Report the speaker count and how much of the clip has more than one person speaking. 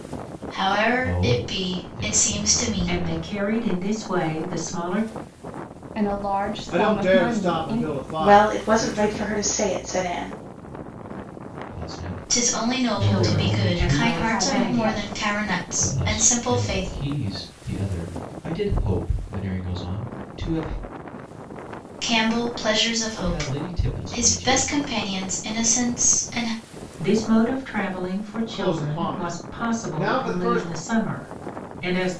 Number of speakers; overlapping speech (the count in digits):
6, about 39%